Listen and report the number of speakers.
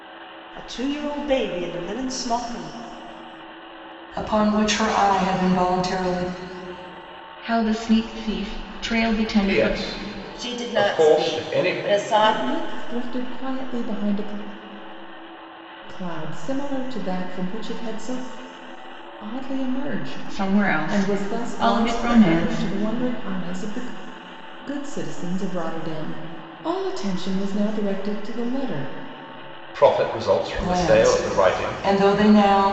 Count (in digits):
6